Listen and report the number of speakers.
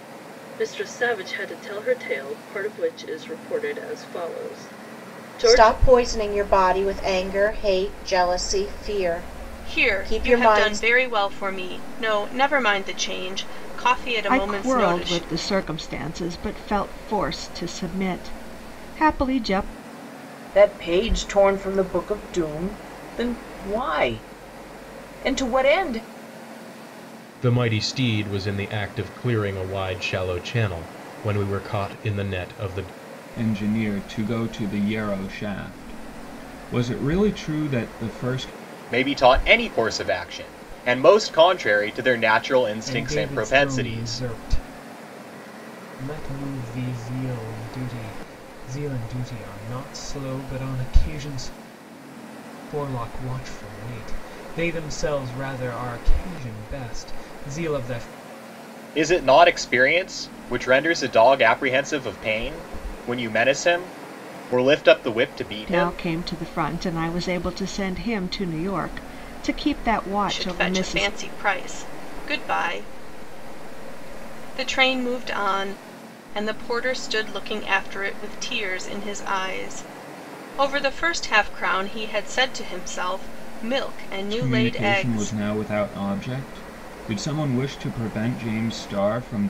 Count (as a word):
nine